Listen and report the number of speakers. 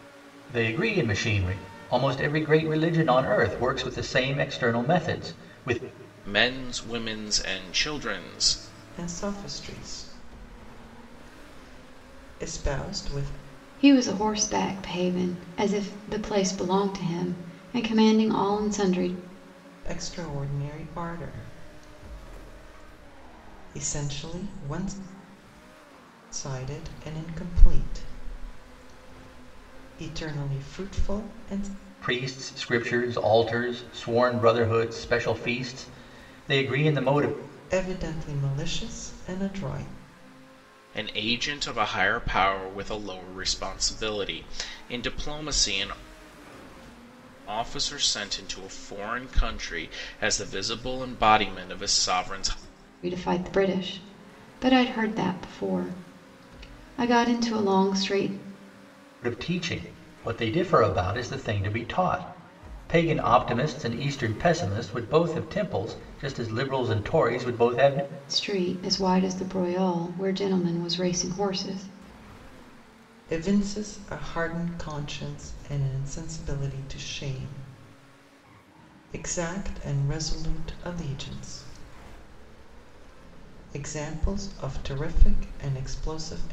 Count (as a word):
four